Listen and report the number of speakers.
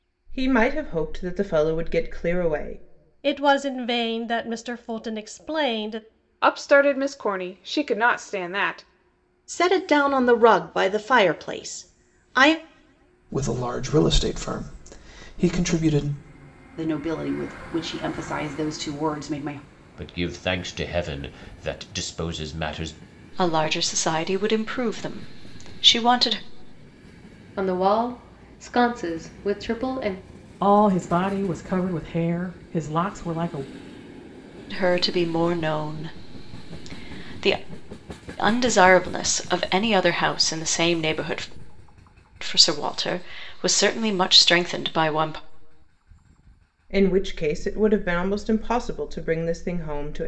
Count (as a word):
ten